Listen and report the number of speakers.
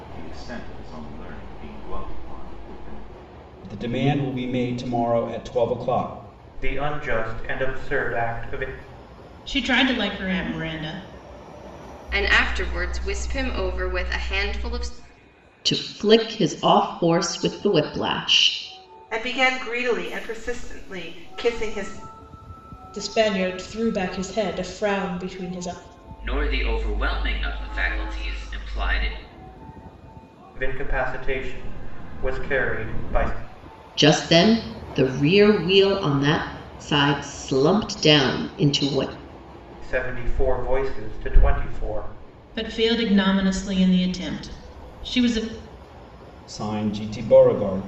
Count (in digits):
9